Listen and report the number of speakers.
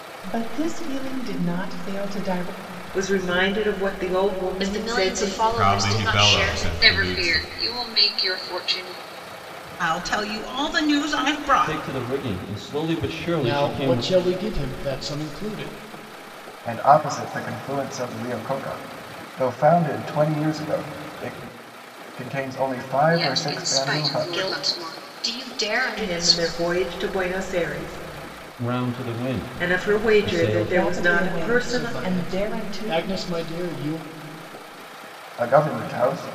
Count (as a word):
nine